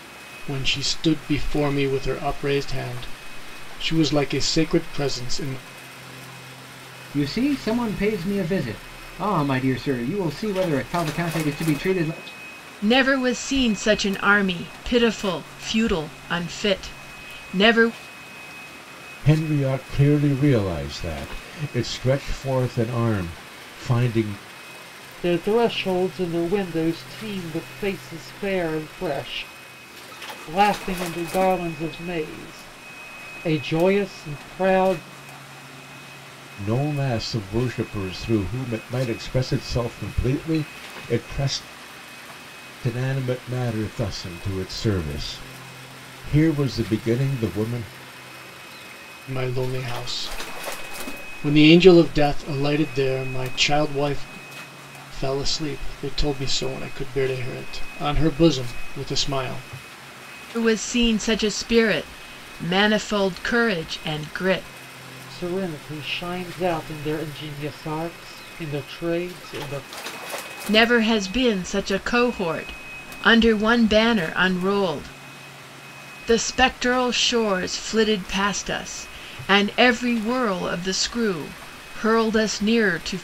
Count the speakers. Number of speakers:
5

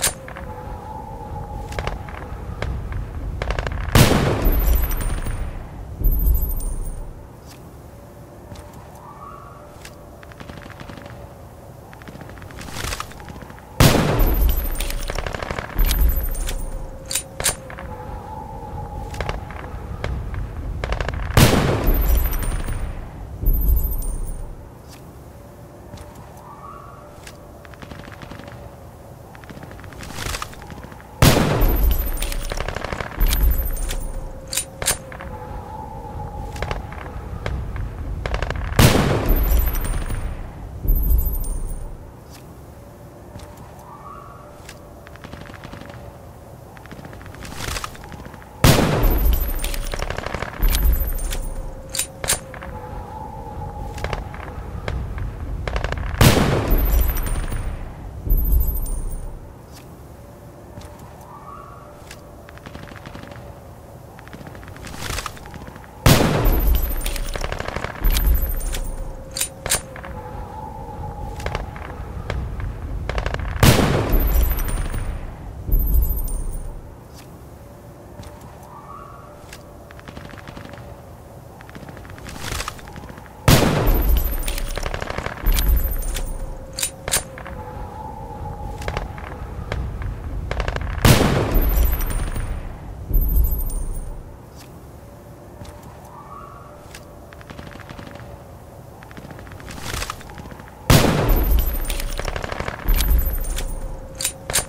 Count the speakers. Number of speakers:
0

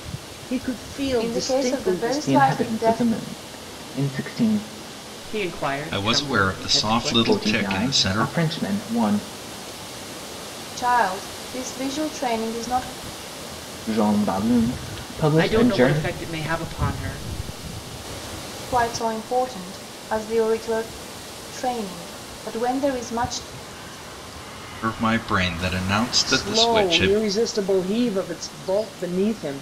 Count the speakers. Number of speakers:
5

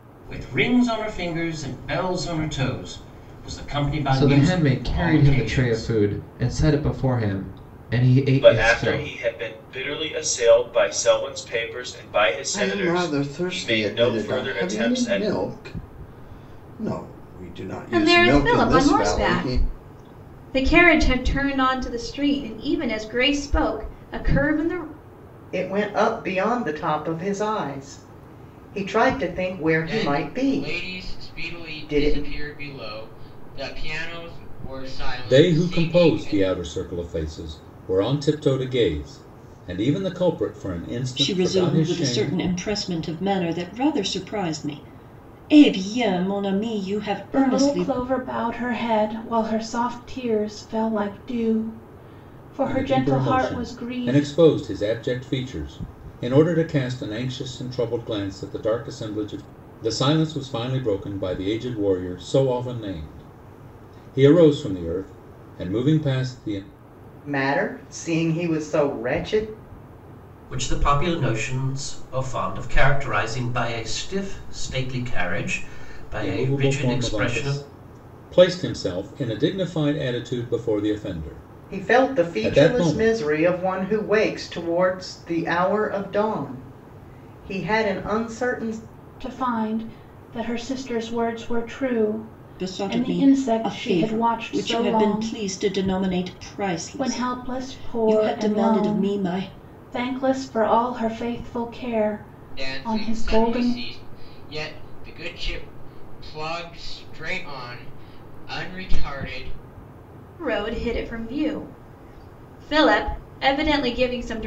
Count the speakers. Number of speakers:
10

